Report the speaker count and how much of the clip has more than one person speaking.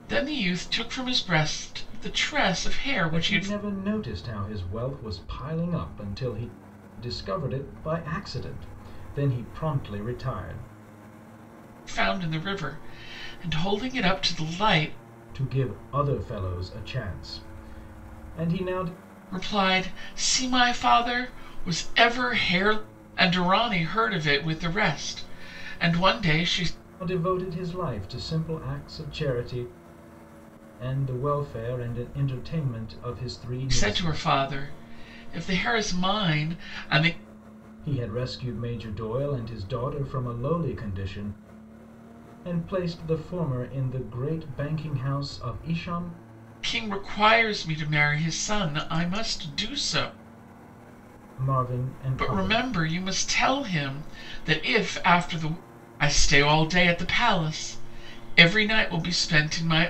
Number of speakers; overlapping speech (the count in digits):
2, about 3%